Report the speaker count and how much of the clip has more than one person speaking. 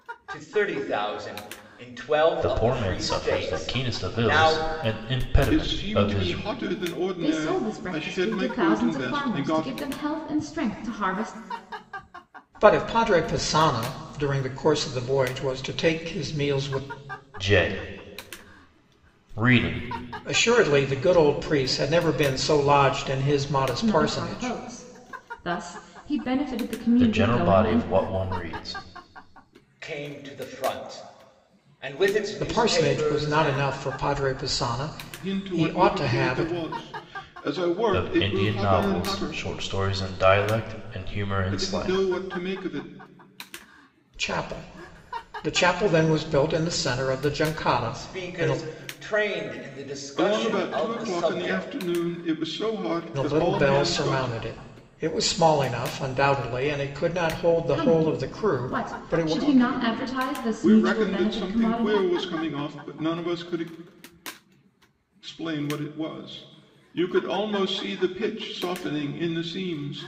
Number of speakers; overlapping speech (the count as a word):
five, about 29%